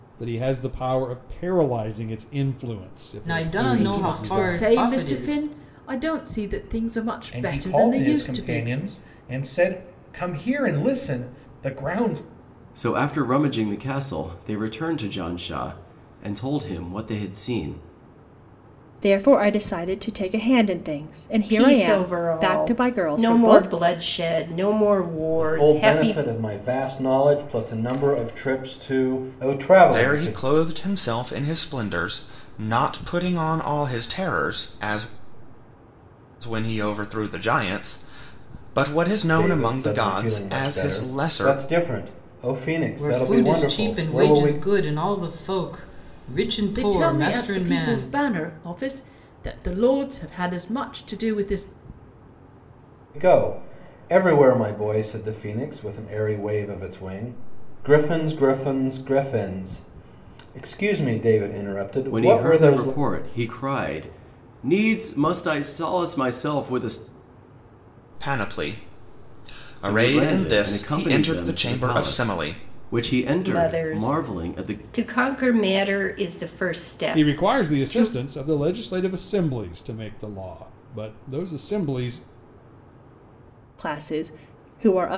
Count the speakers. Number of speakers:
nine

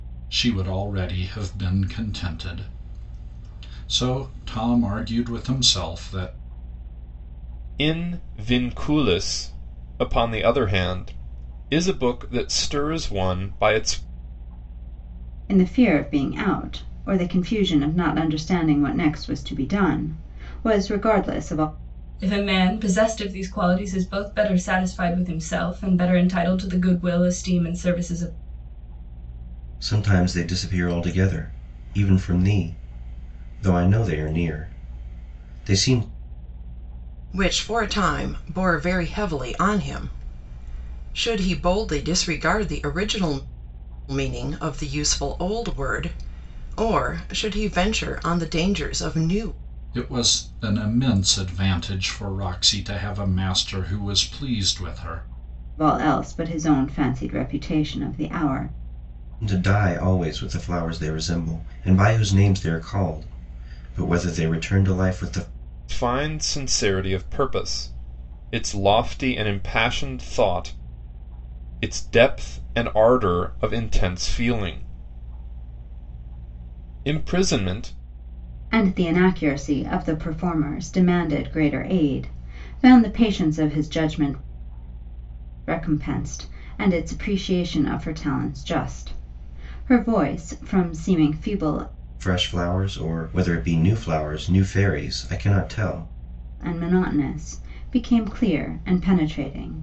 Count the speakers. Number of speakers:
six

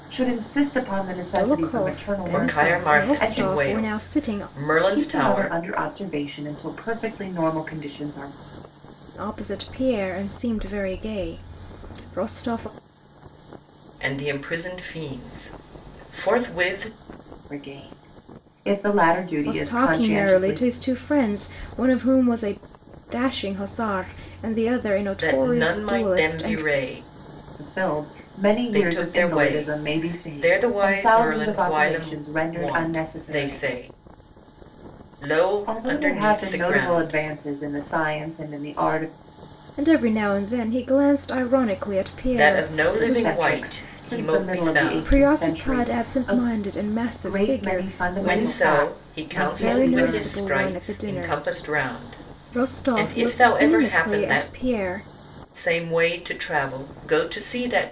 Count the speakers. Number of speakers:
three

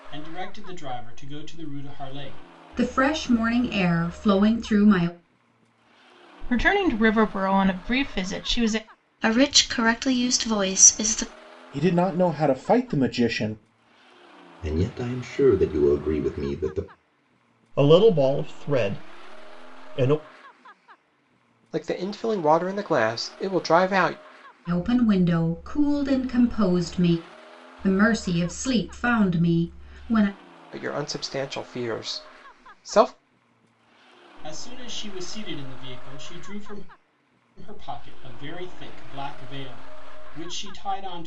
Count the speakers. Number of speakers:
eight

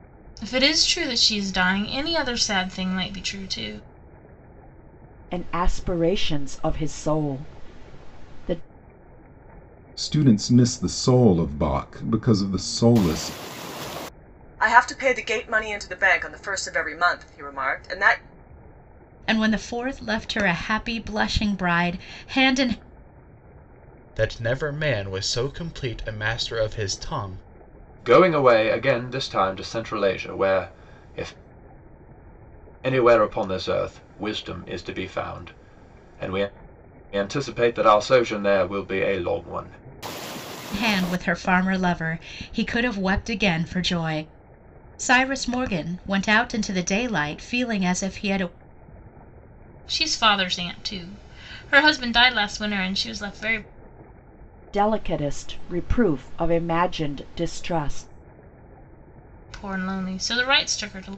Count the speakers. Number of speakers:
seven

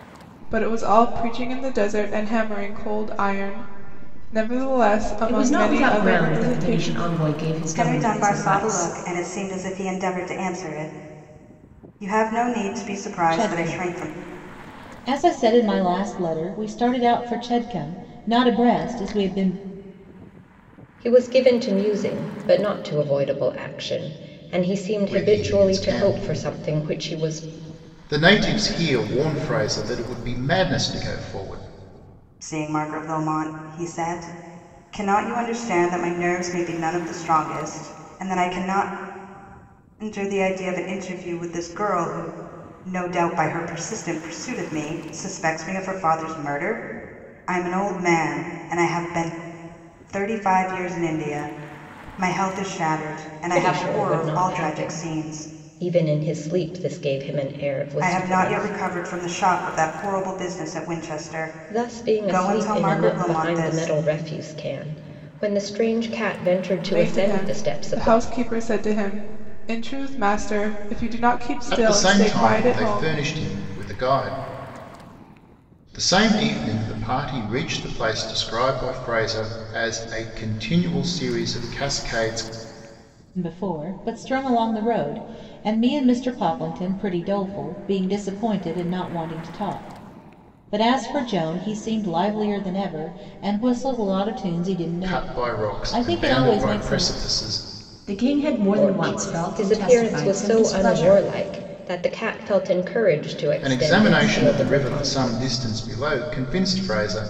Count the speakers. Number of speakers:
six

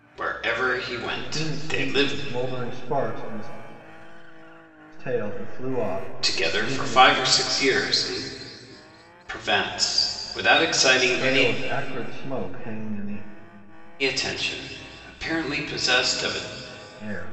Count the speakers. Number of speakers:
two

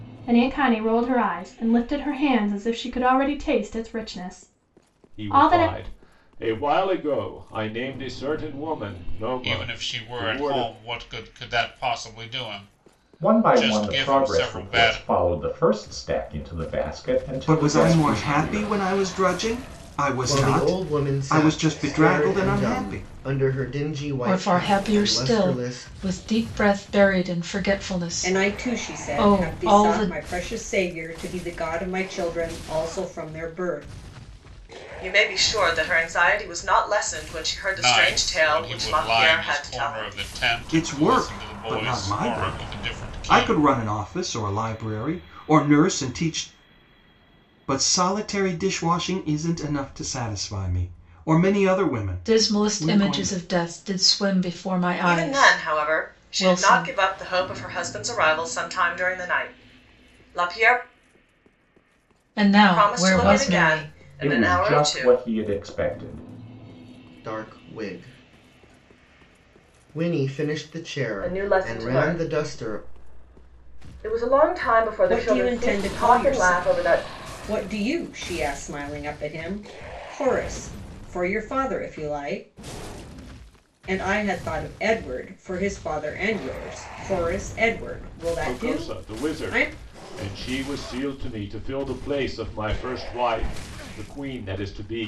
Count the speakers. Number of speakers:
nine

